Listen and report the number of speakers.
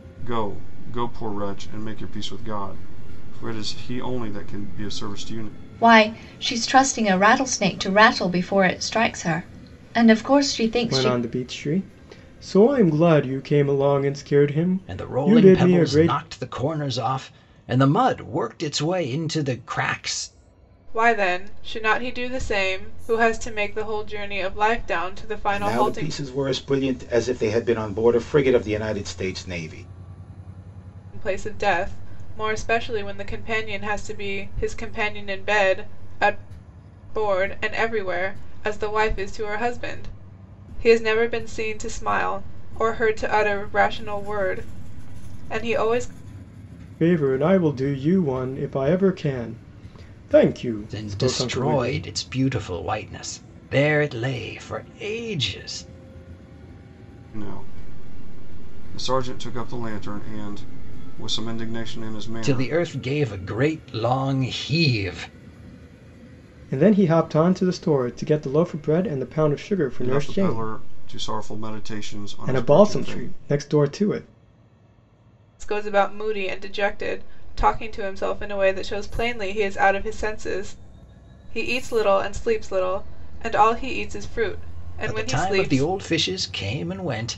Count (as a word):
six